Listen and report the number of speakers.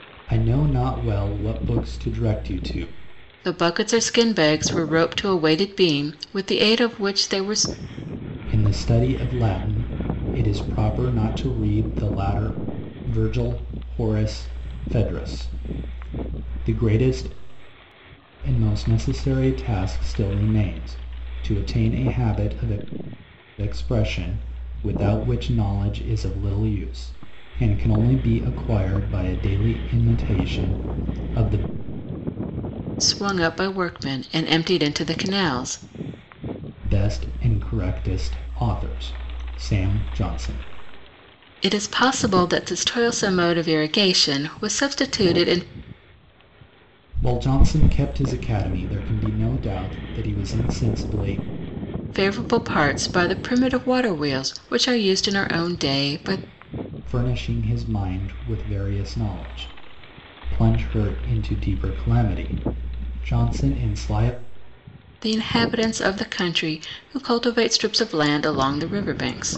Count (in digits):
2